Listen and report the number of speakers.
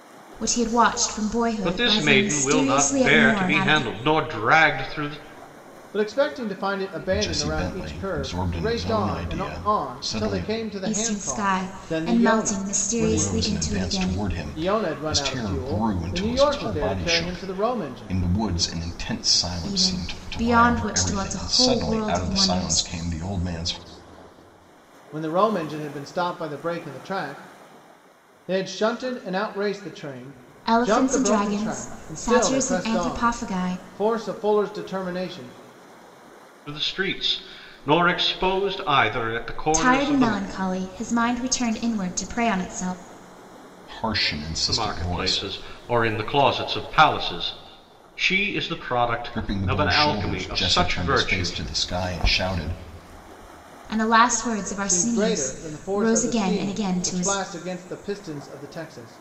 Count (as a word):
four